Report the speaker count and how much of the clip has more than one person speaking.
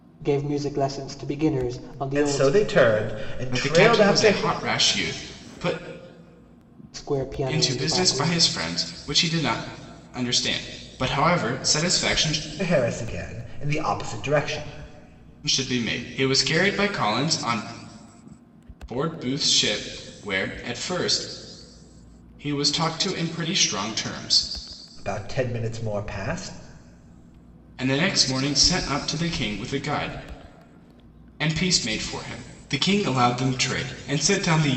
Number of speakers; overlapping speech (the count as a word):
three, about 7%